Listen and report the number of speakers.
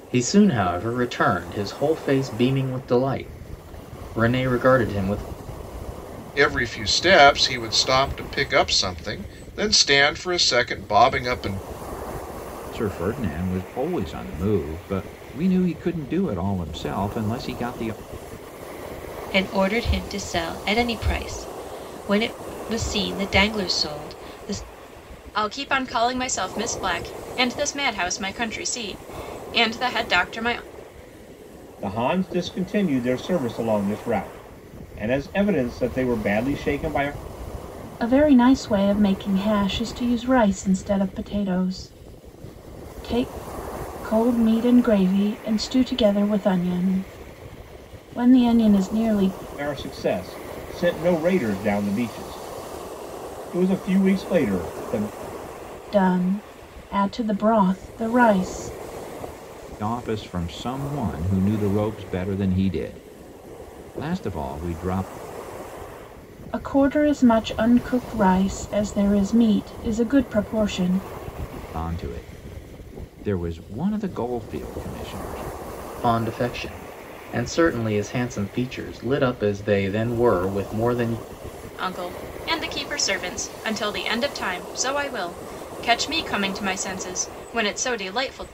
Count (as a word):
seven